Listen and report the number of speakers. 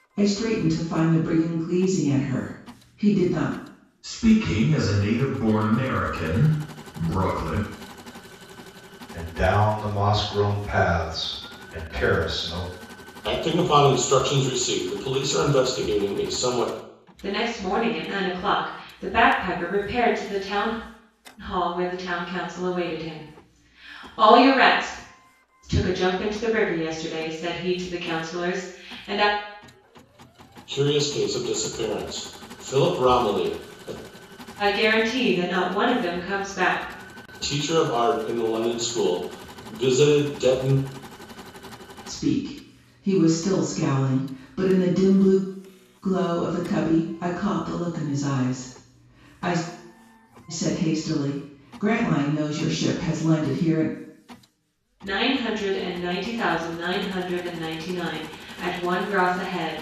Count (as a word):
five